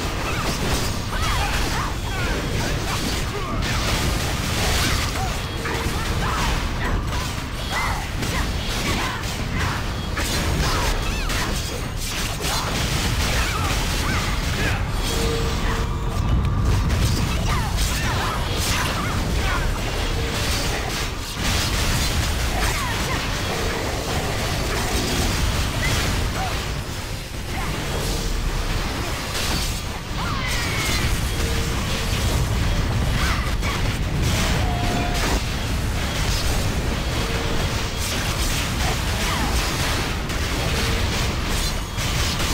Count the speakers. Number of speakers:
zero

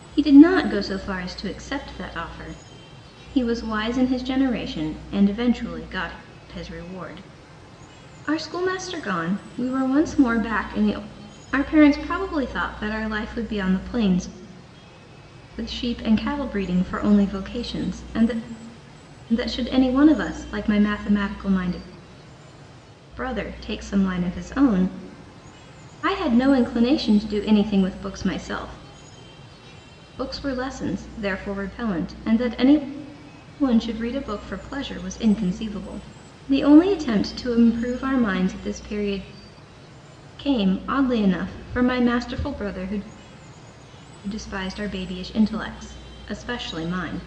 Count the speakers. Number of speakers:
one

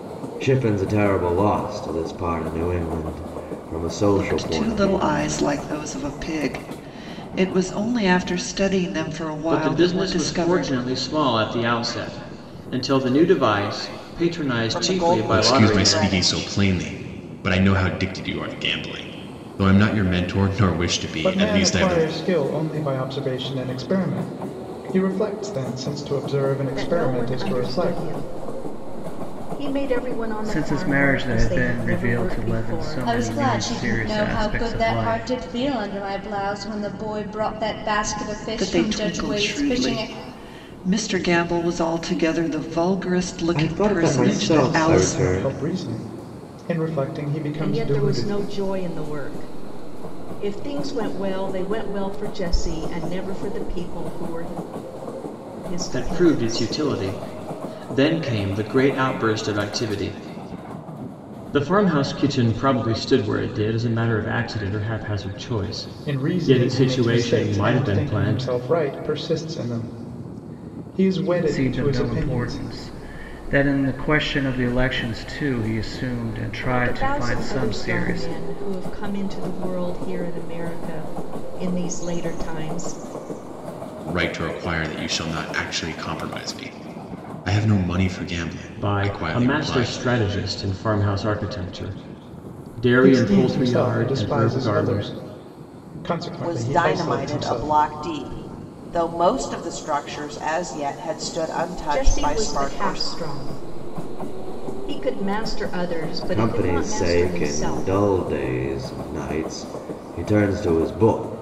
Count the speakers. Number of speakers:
nine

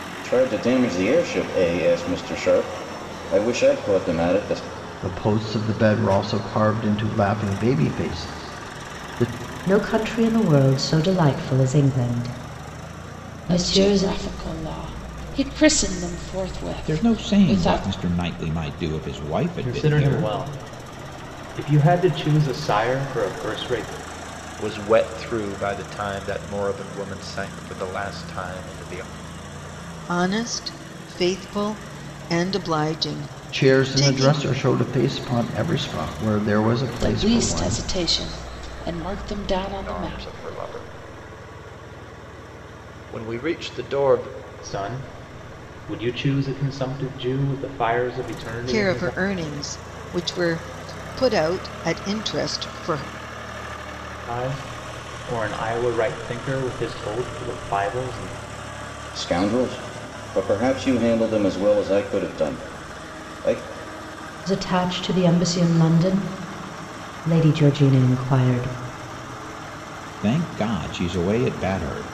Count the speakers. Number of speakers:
eight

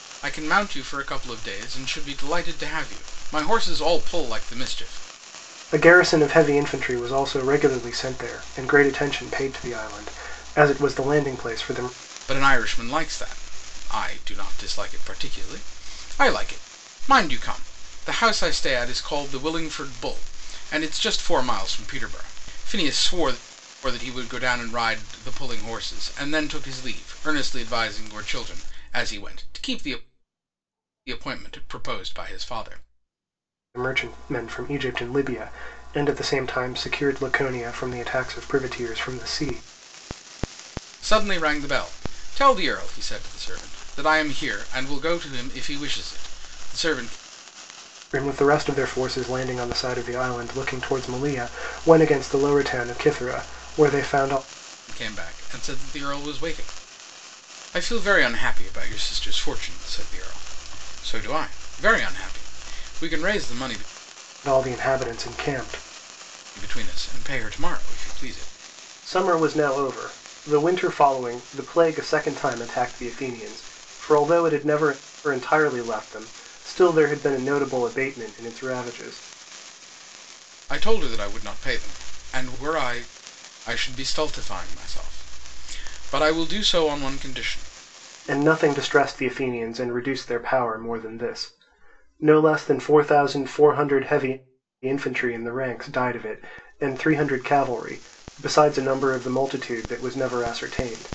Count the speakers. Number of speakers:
two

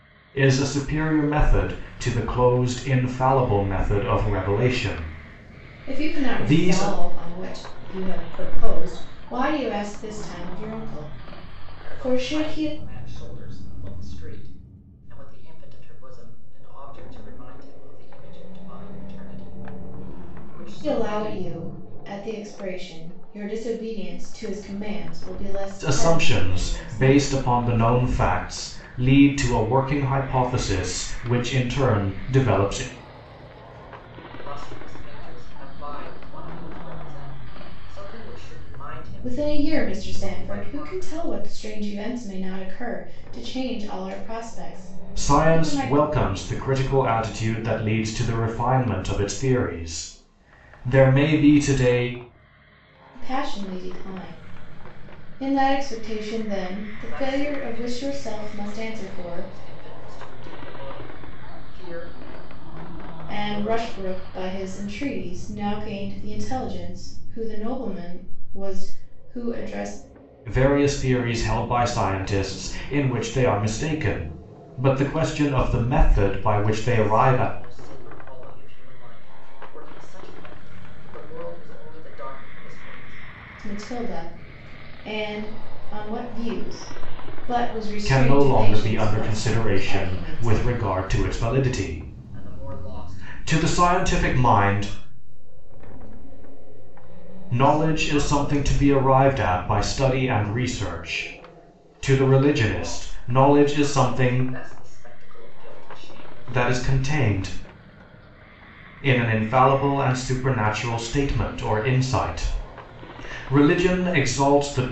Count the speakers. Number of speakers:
three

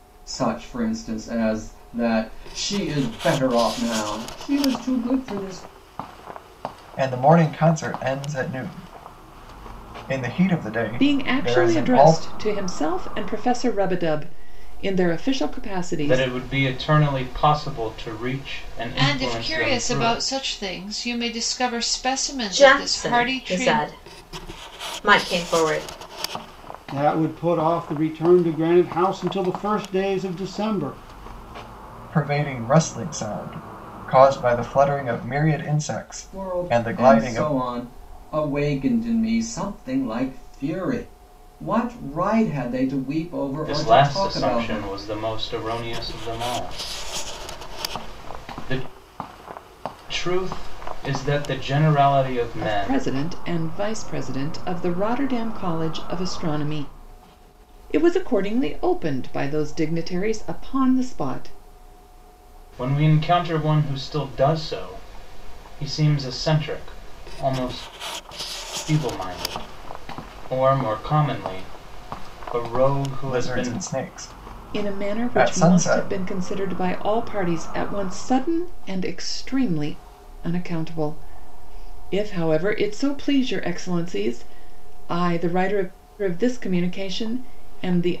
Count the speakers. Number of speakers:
seven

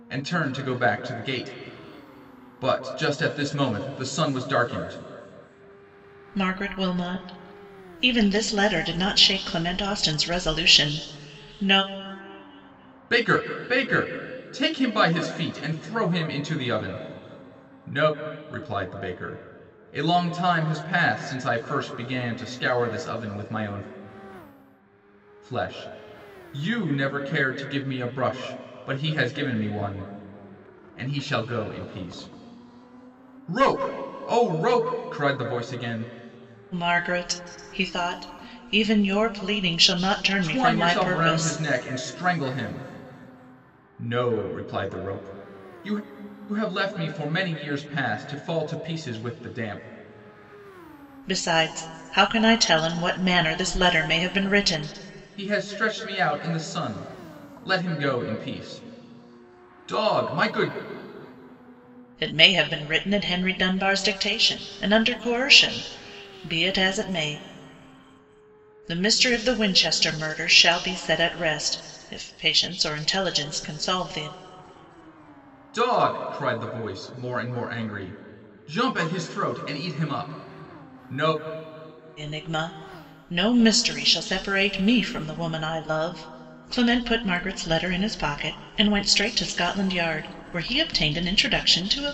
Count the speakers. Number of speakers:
two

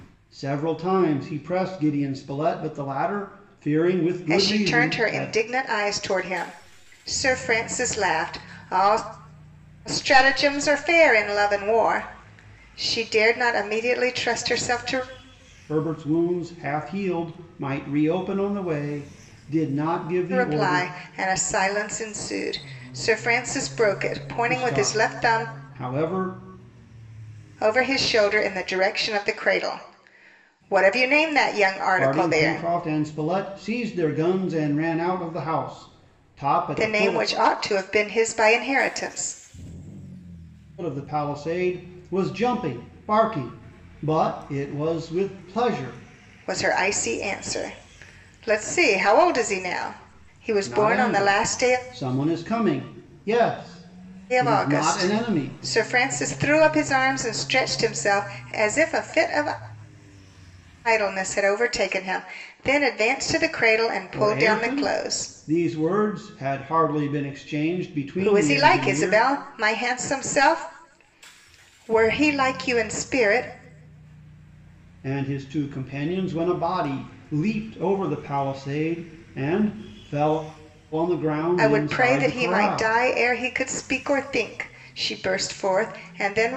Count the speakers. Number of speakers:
two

